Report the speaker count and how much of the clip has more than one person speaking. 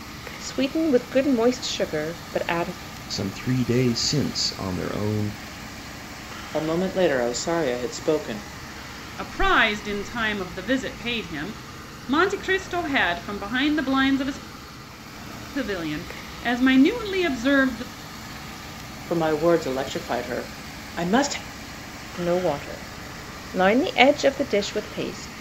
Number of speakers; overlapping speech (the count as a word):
four, no overlap